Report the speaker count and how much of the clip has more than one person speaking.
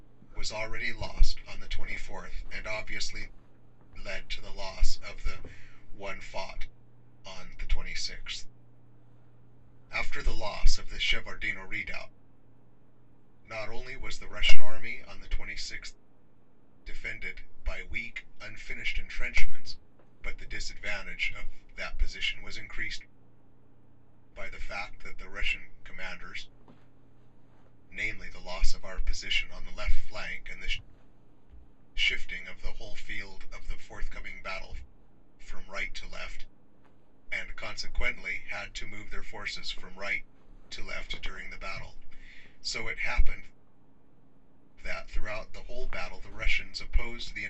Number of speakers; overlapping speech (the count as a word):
one, no overlap